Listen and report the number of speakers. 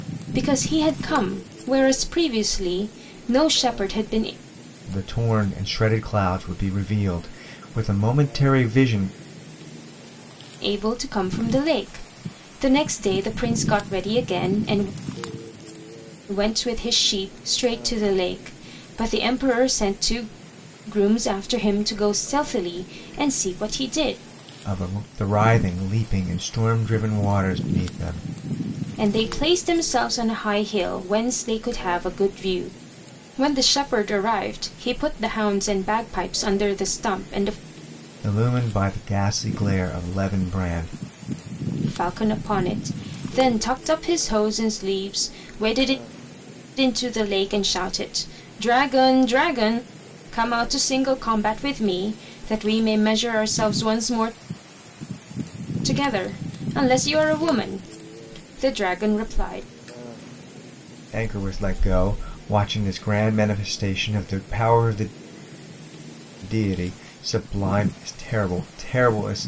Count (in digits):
2